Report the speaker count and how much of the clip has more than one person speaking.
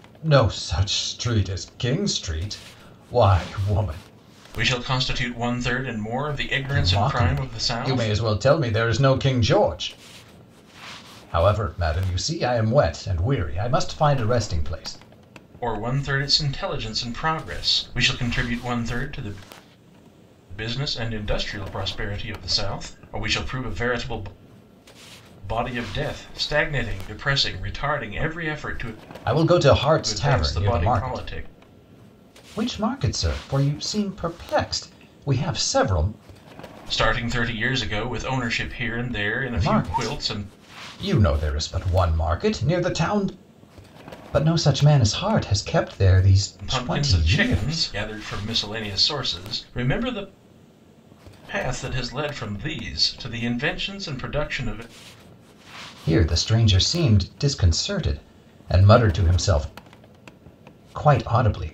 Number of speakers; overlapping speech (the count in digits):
2, about 8%